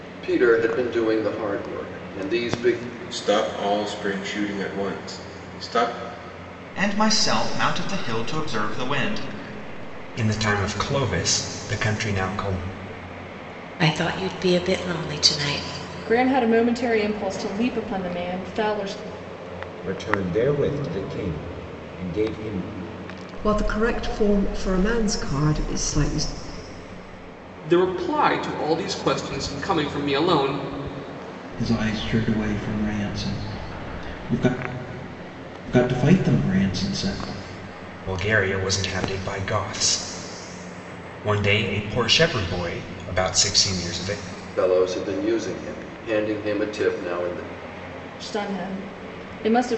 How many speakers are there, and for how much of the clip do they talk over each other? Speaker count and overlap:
10, no overlap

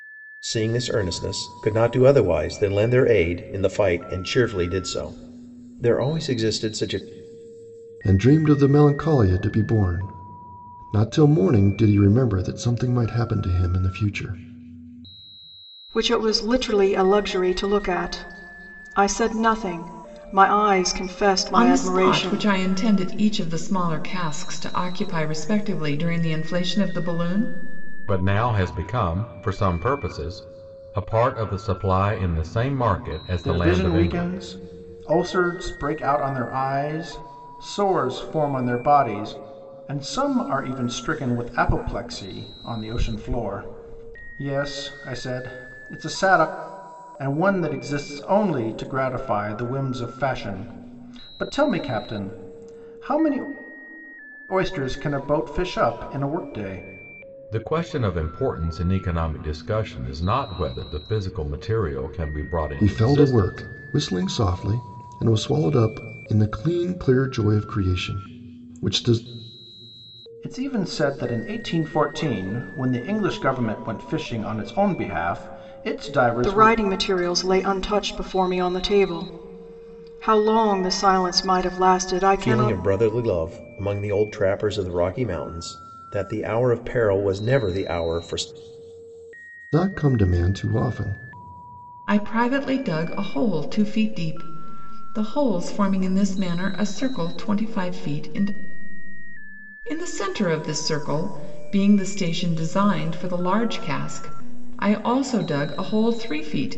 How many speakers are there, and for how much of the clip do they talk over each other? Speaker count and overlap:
6, about 4%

